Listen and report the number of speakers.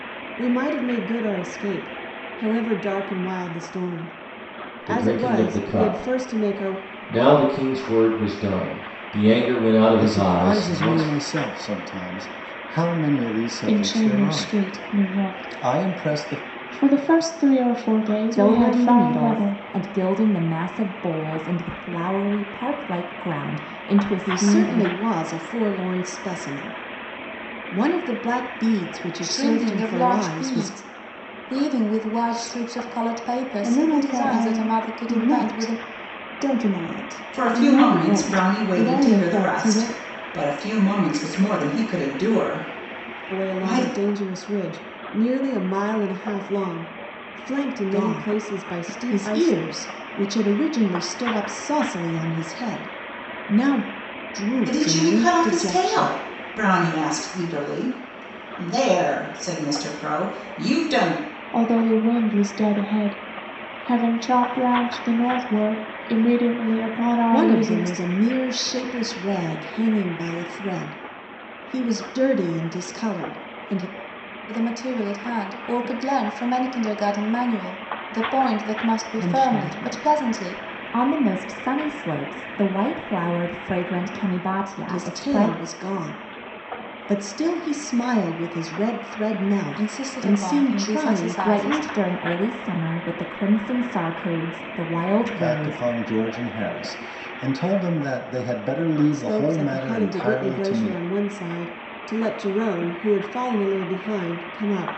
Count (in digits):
9